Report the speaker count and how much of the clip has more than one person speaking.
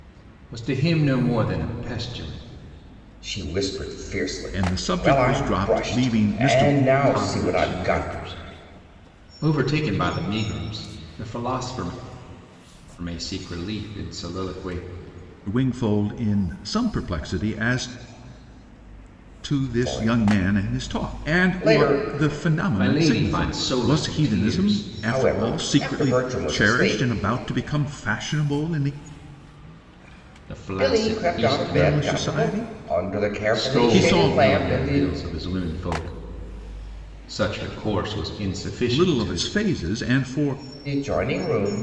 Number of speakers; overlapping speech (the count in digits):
3, about 34%